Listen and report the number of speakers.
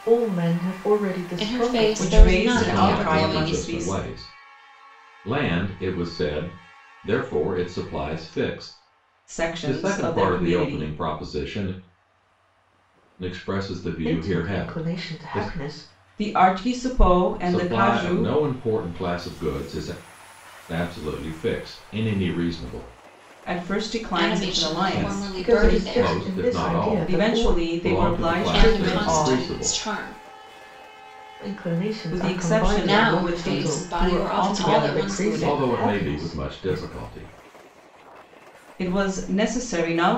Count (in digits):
4